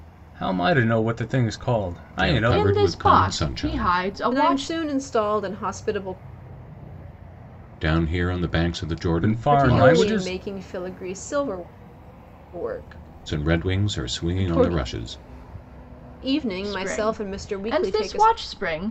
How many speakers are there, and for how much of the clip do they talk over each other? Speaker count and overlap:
4, about 36%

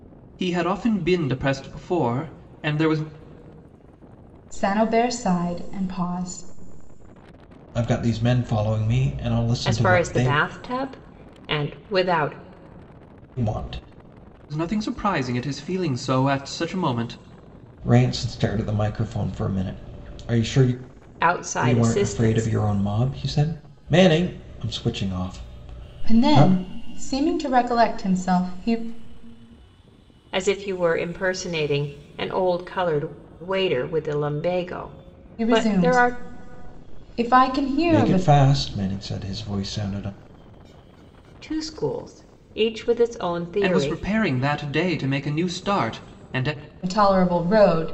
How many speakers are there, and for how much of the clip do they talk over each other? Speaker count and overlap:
4, about 8%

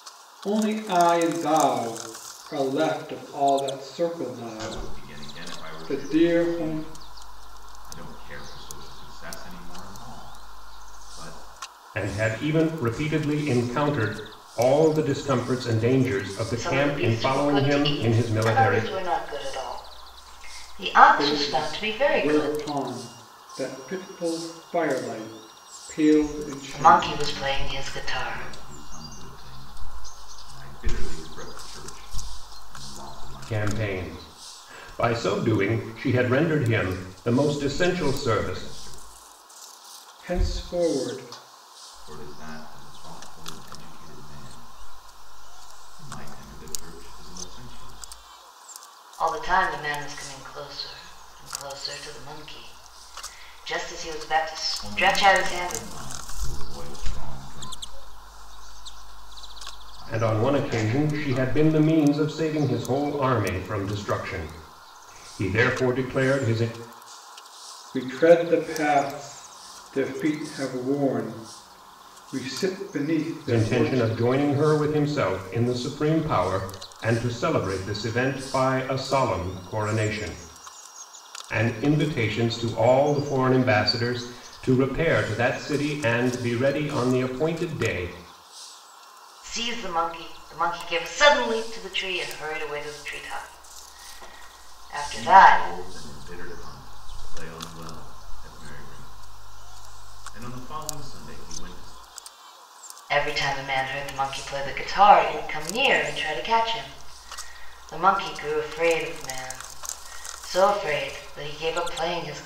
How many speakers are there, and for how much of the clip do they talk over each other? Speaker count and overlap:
4, about 12%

